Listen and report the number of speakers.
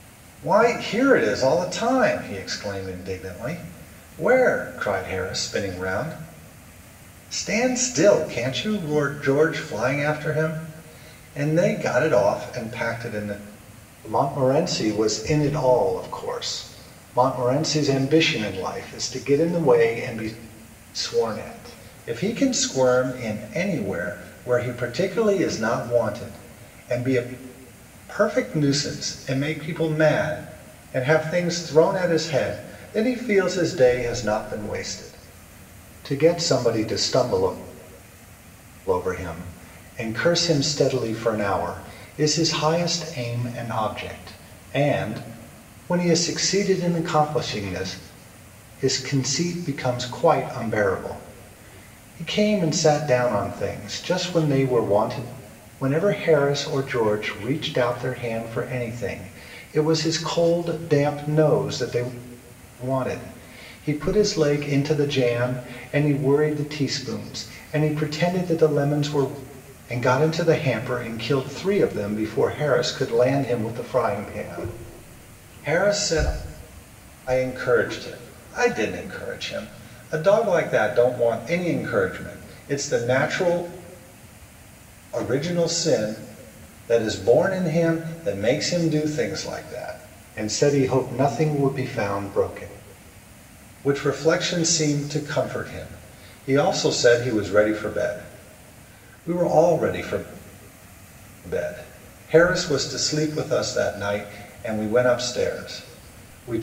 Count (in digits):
1